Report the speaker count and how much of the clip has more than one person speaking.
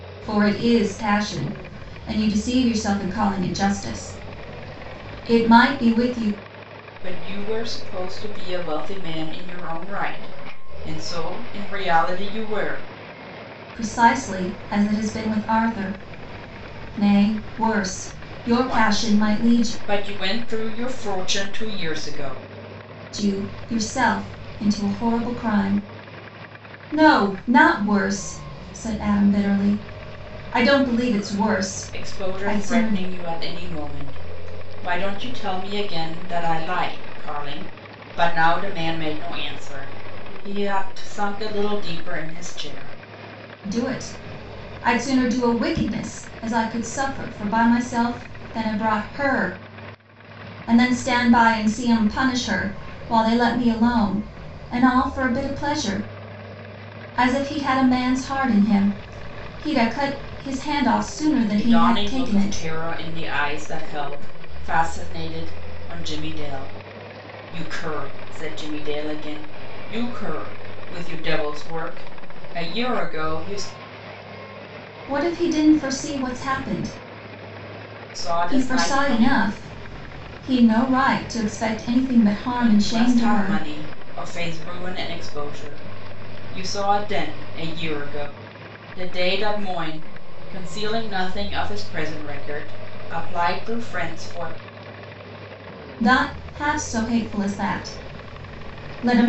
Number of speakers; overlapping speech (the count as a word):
two, about 6%